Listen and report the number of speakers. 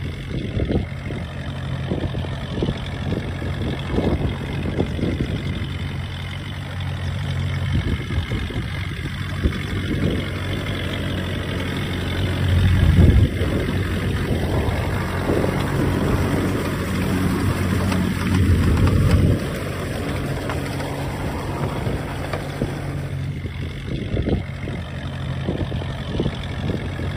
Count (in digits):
0